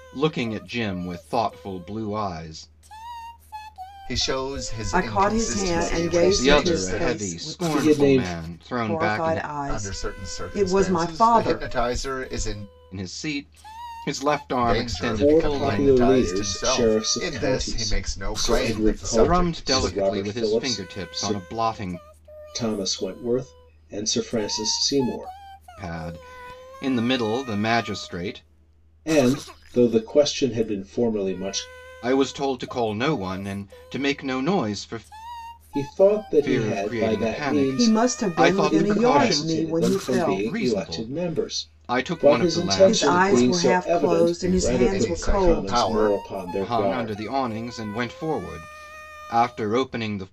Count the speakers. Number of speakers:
4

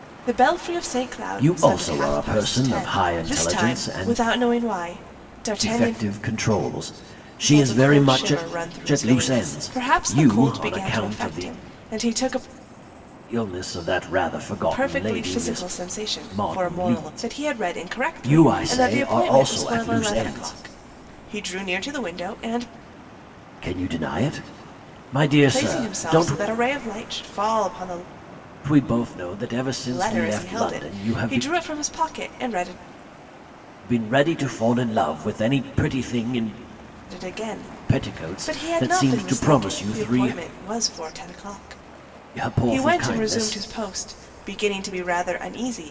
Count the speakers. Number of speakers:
2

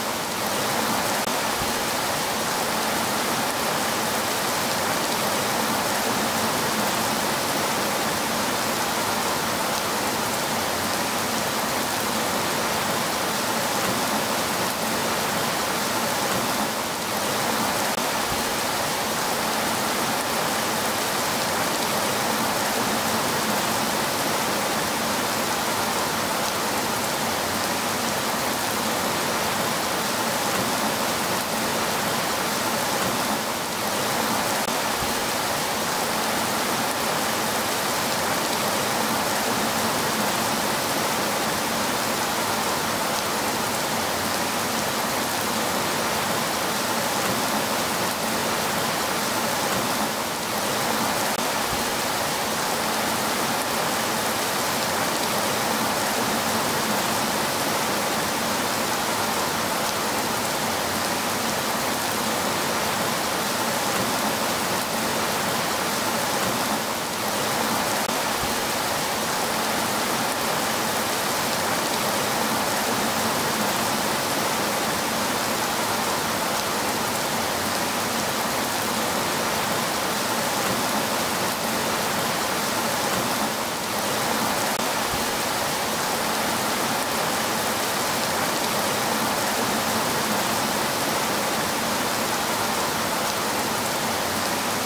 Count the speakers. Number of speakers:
0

